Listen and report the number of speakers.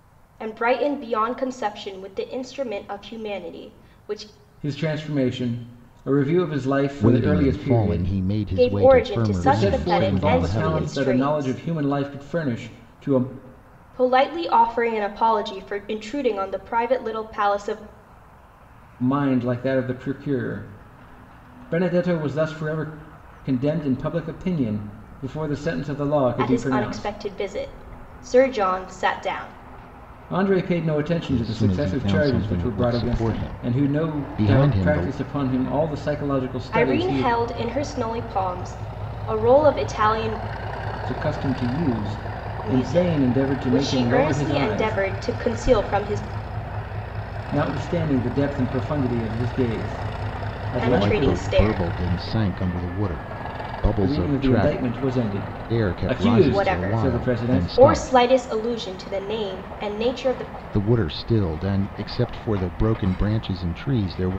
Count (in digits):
3